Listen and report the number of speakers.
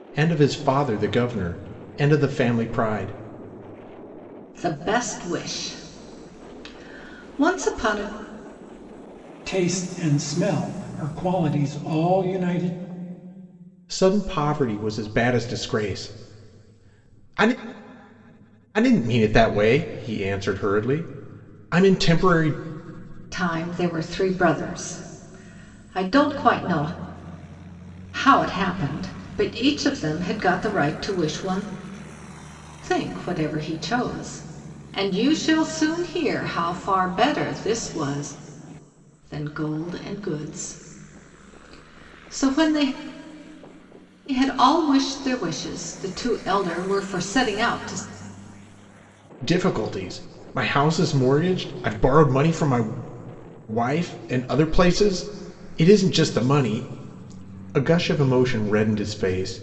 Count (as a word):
three